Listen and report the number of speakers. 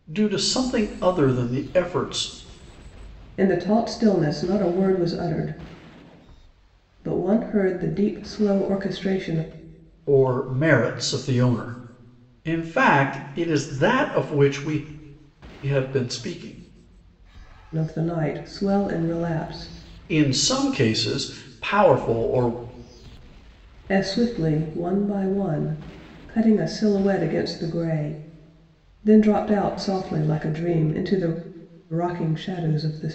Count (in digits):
2